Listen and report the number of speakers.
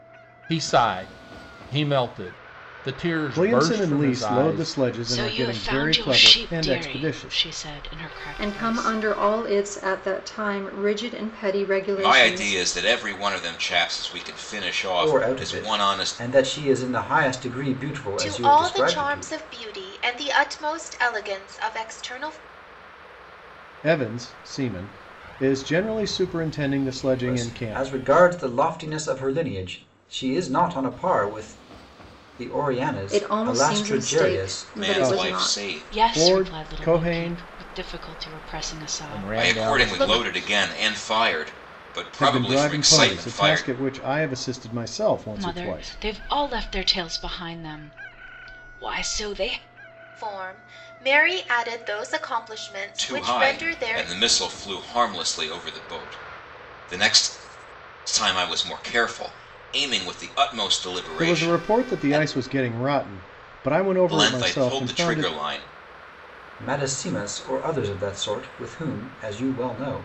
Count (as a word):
seven